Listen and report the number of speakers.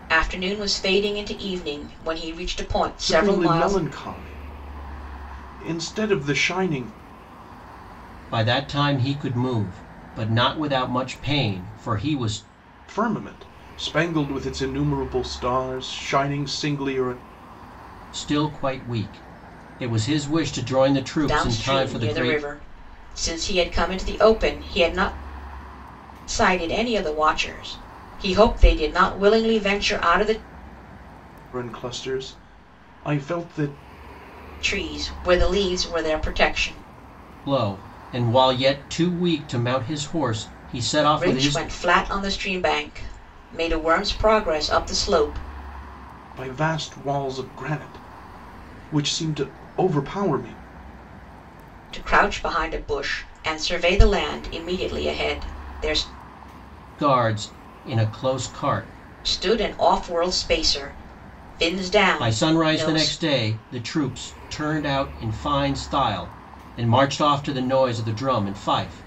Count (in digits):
3